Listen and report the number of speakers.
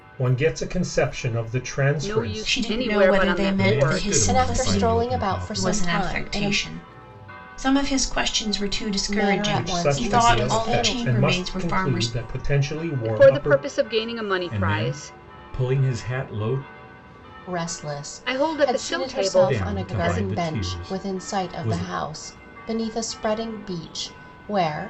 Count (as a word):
five